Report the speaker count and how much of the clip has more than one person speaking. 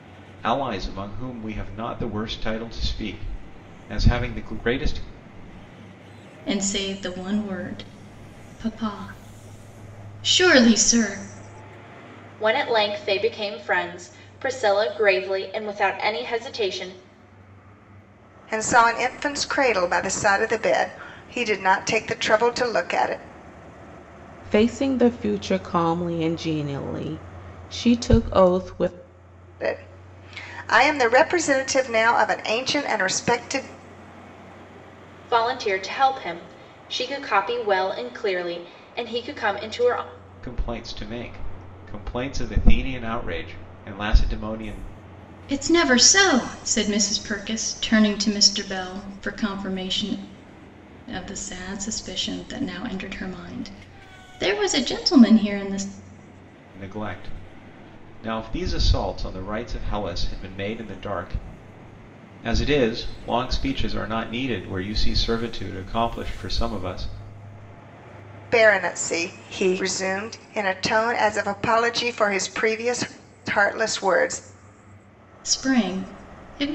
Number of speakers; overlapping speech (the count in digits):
5, no overlap